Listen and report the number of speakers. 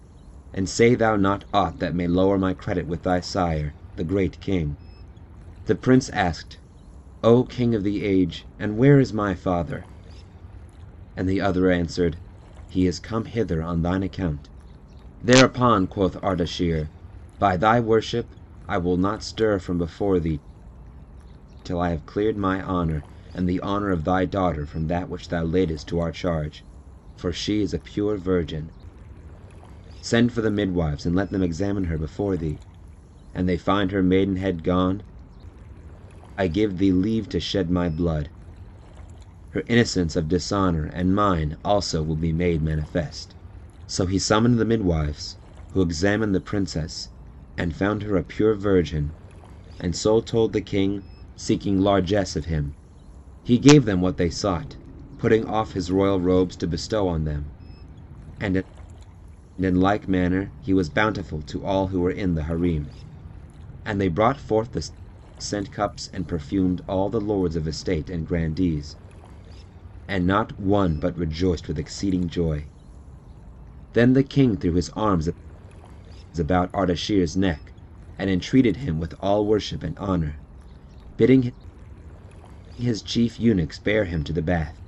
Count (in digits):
1